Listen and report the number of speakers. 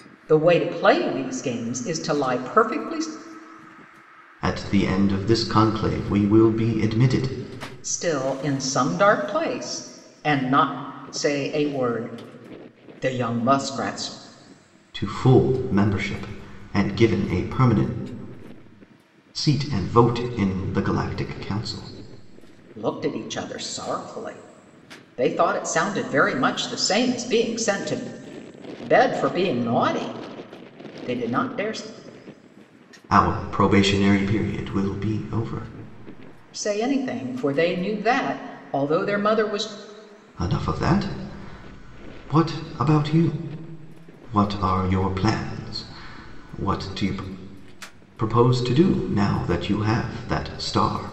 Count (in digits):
2